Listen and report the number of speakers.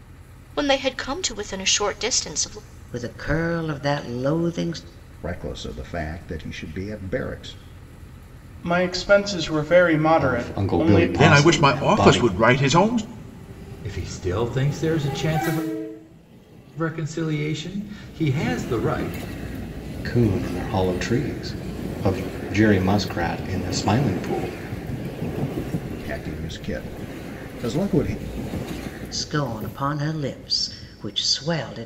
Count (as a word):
seven